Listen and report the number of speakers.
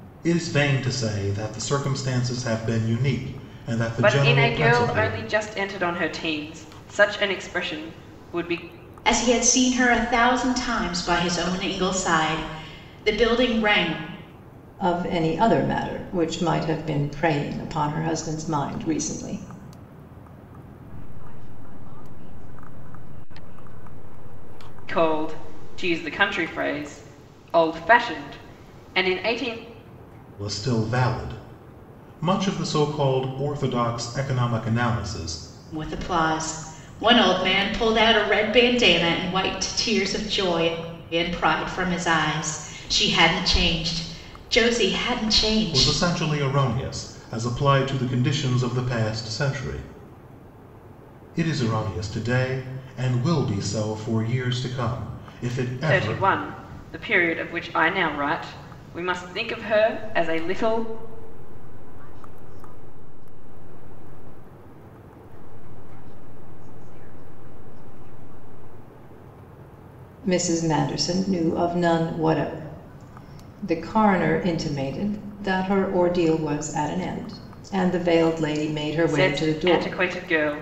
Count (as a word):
five